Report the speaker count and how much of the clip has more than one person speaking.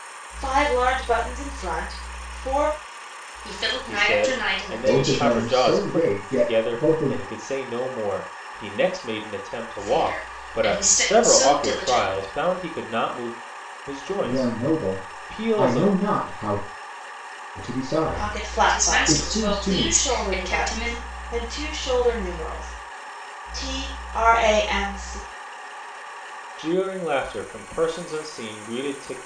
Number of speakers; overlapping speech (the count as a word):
four, about 36%